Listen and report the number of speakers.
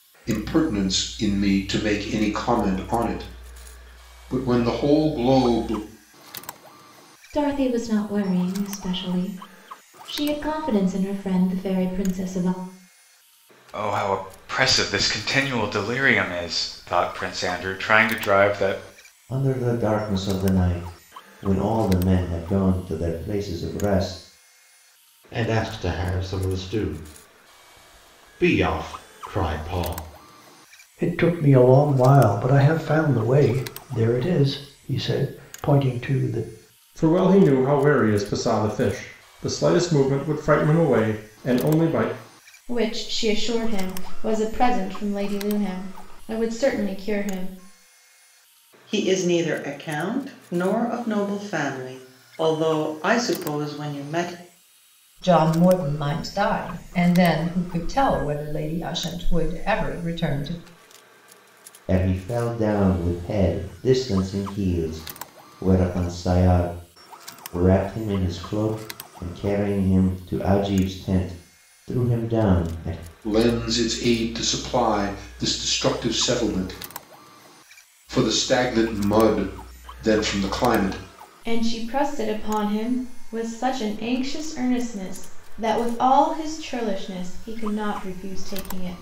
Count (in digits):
10